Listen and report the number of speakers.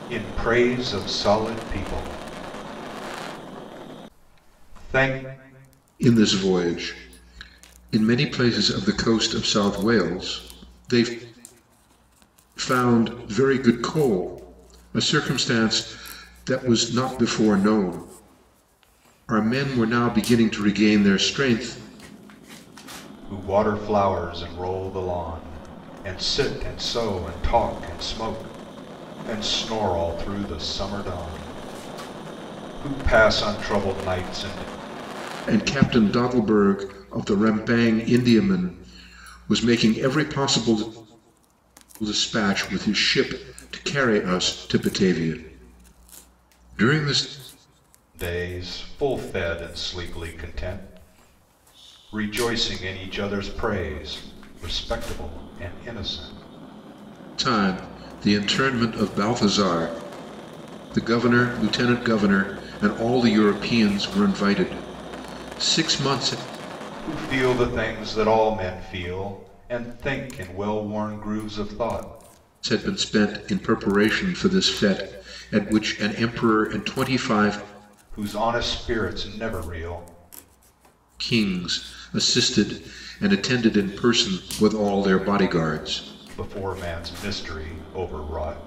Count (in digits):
2